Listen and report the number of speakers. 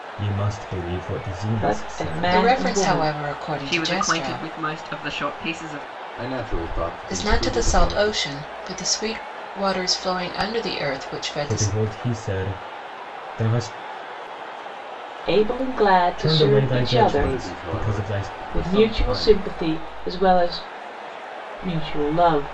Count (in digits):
5